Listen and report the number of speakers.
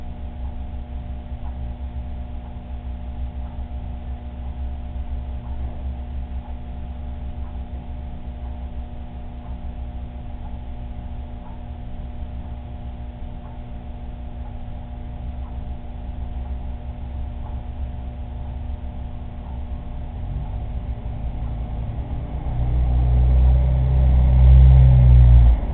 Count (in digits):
0